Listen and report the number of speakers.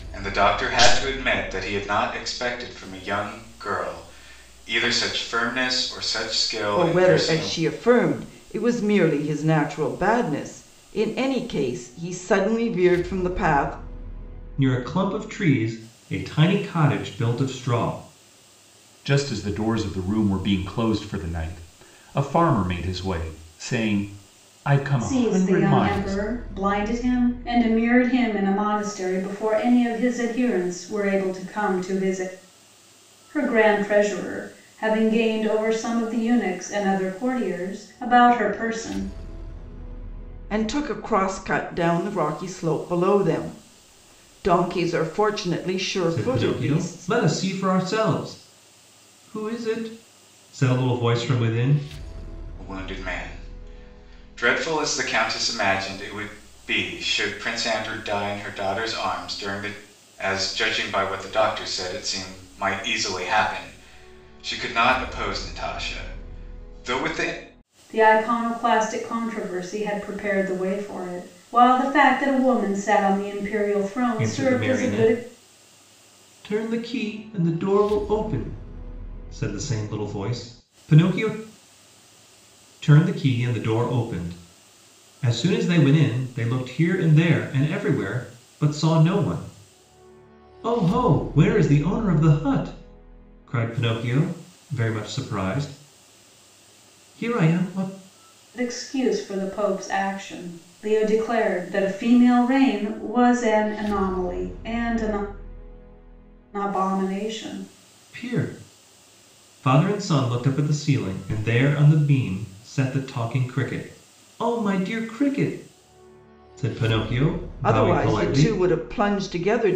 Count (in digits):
5